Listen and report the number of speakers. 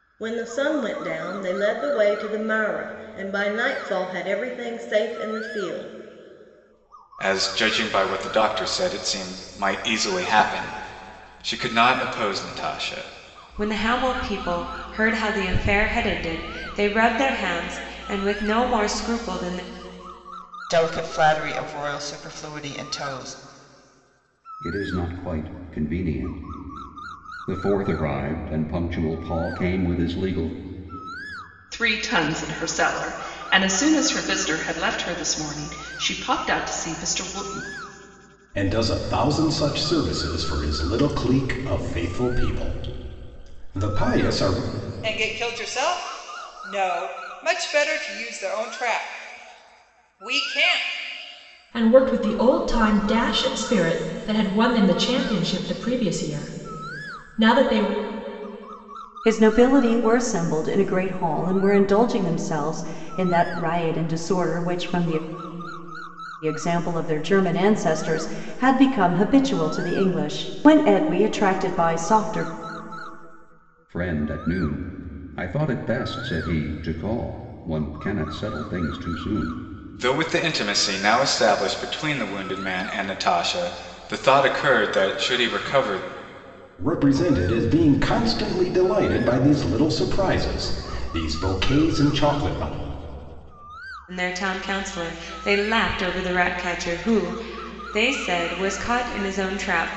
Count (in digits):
10